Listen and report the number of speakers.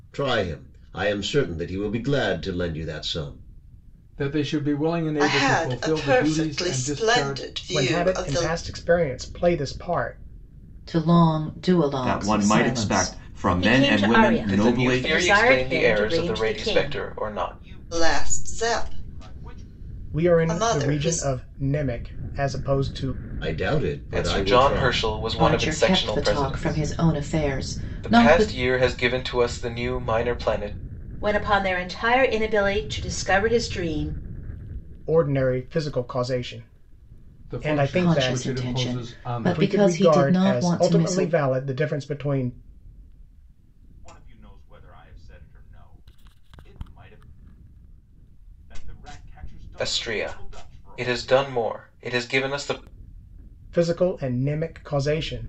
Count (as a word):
nine